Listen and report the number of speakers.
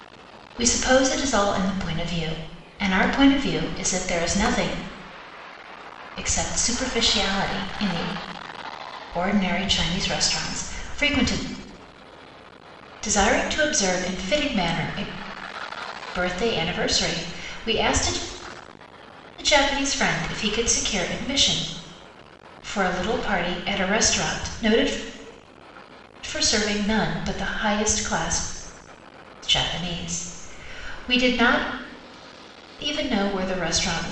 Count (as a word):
one